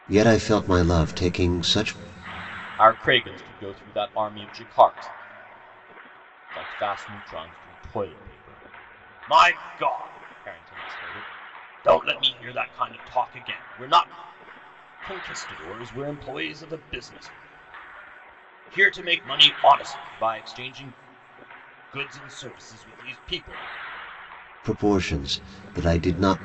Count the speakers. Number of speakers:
2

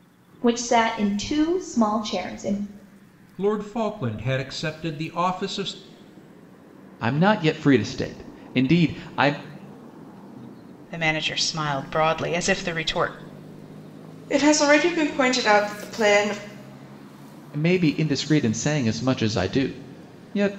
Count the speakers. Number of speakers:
5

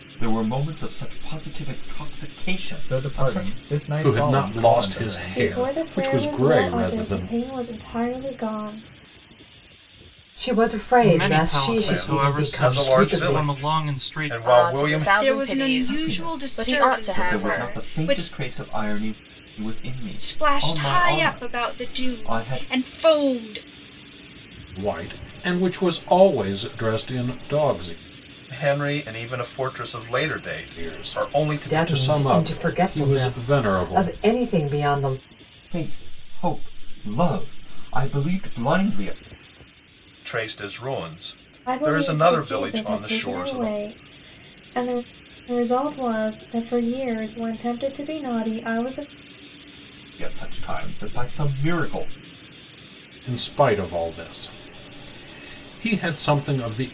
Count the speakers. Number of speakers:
9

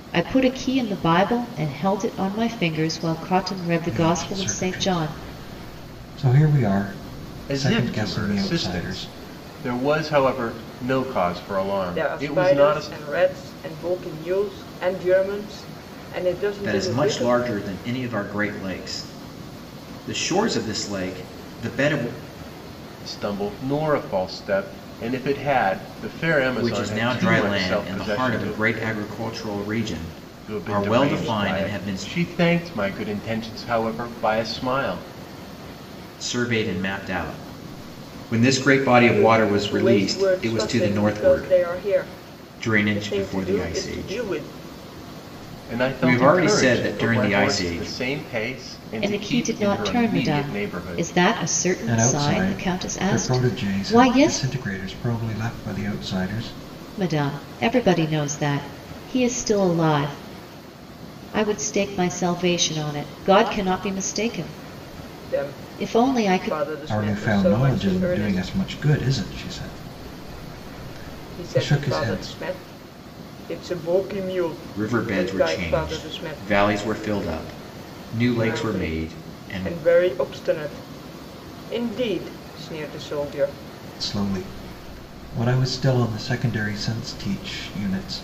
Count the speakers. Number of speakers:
5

